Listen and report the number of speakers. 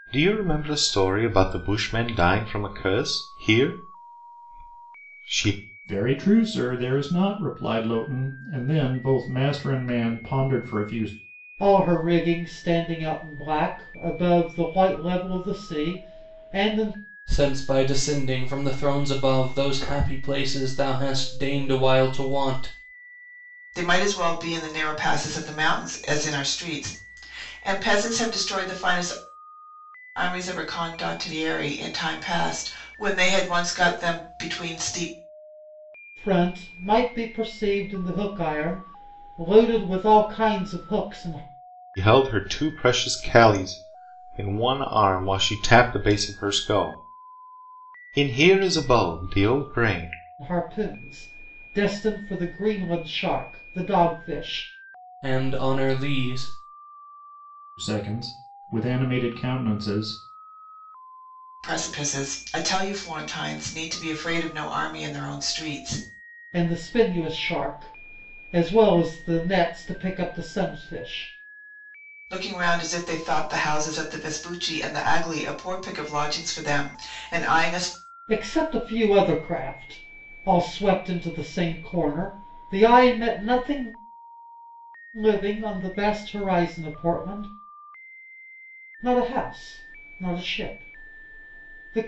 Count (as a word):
five